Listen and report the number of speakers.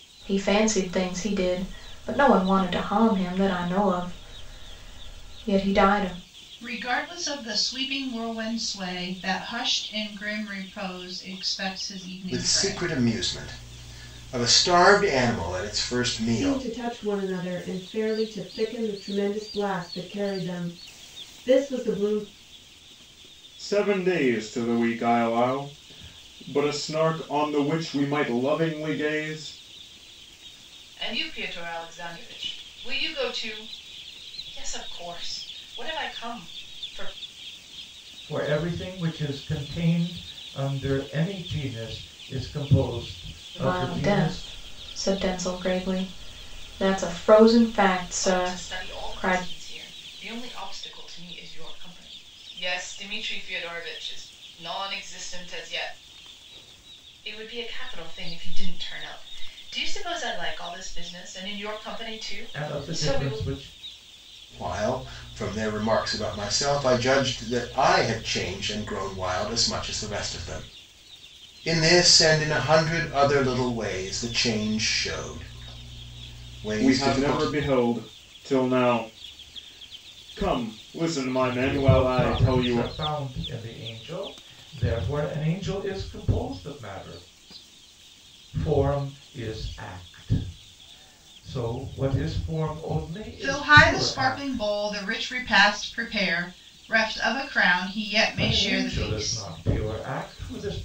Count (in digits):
7